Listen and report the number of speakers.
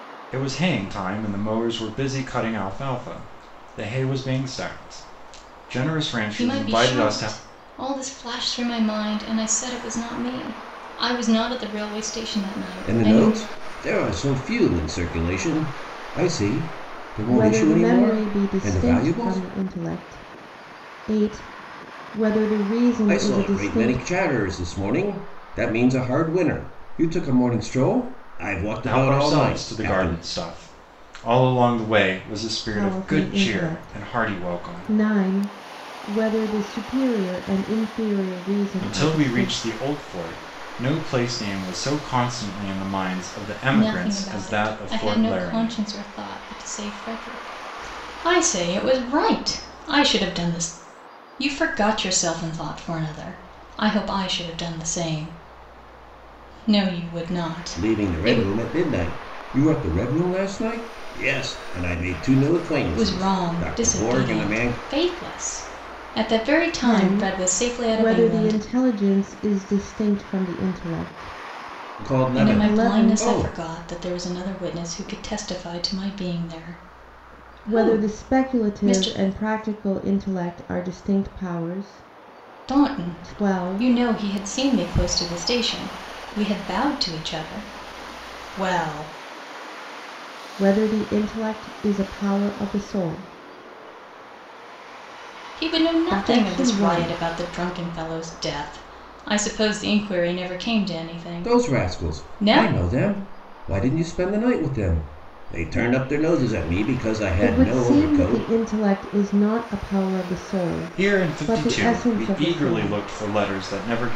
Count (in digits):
4